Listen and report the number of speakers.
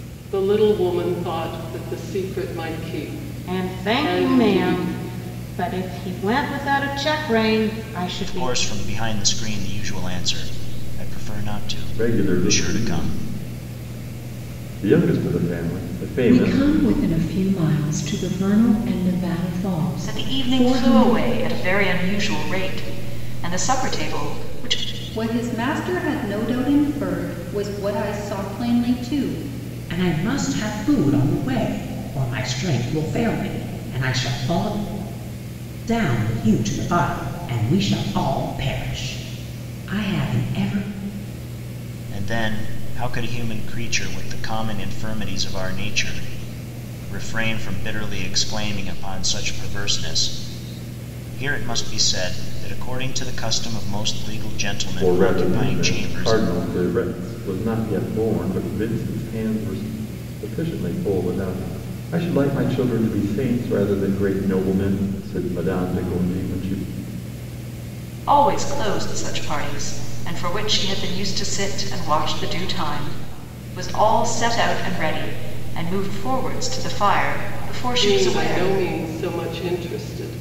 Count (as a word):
eight